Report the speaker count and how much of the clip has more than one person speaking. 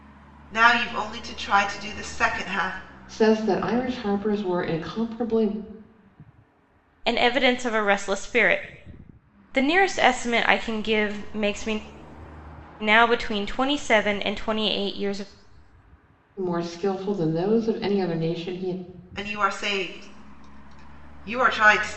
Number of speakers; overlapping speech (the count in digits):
3, no overlap